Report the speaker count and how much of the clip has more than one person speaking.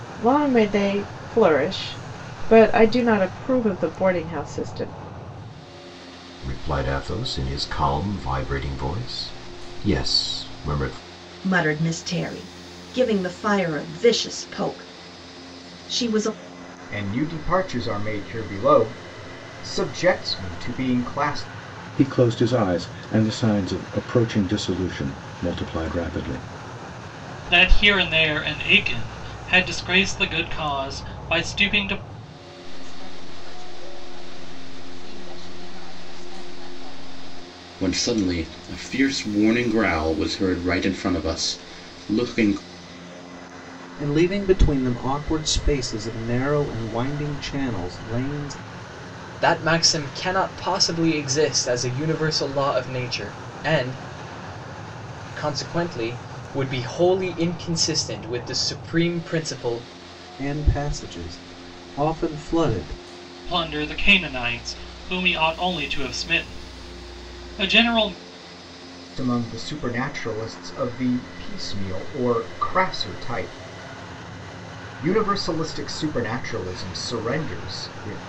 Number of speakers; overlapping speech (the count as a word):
ten, no overlap